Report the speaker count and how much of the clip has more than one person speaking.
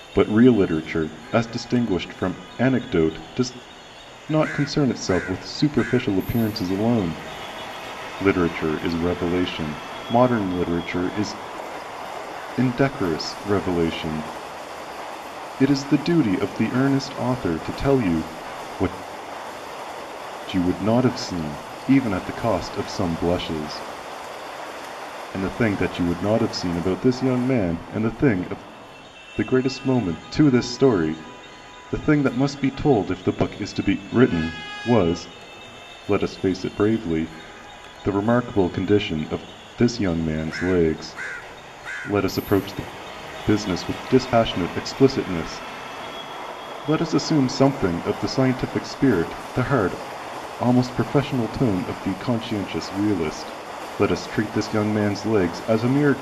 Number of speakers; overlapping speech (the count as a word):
one, no overlap